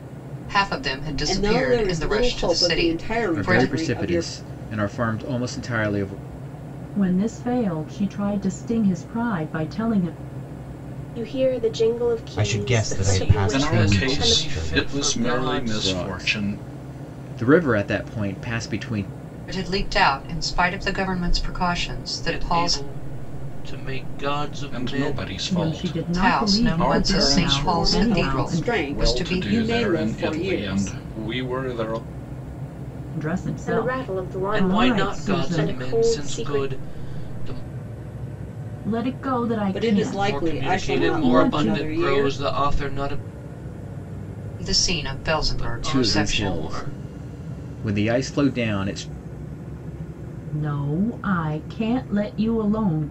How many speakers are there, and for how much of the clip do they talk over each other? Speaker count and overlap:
eight, about 40%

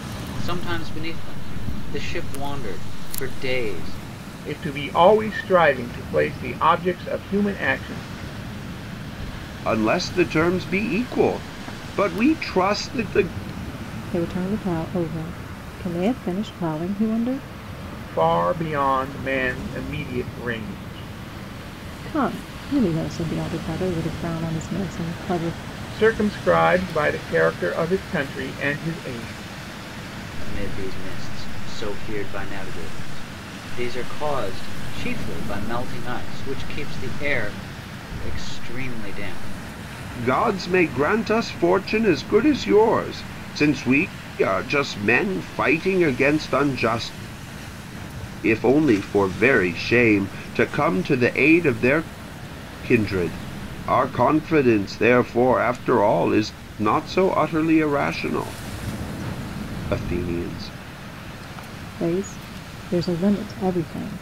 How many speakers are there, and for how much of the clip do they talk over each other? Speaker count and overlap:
four, no overlap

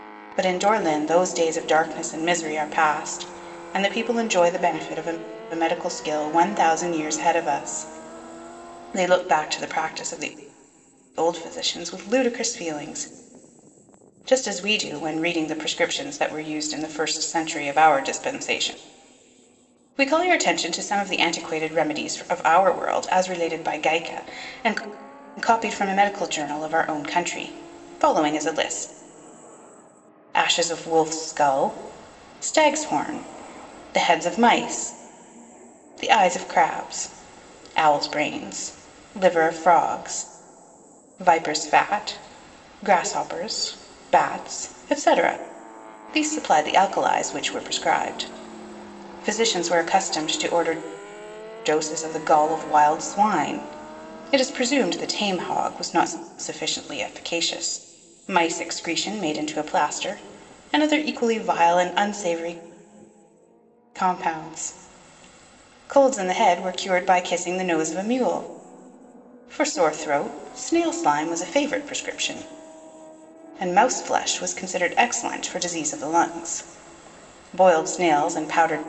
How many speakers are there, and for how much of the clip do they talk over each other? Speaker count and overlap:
one, no overlap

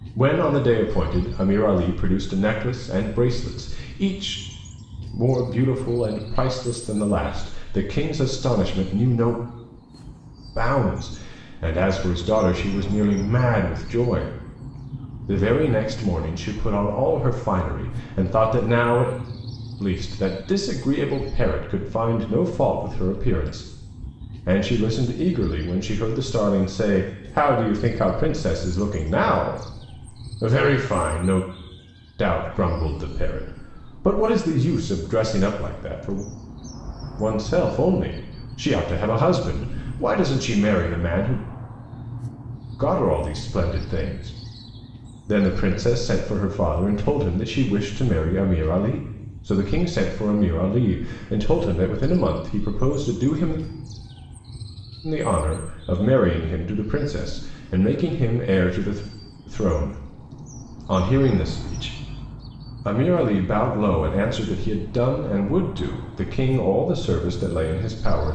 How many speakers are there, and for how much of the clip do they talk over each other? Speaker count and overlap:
one, no overlap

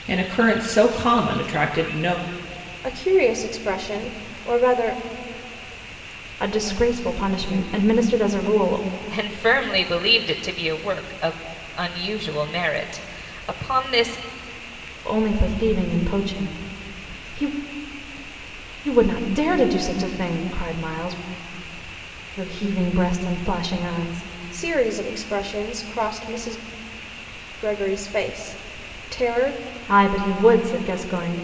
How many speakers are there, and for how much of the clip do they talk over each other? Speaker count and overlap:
four, no overlap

